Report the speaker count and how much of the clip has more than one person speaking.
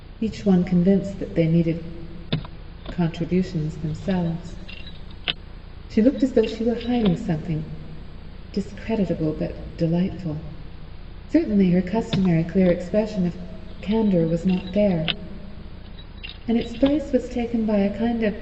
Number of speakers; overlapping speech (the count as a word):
one, no overlap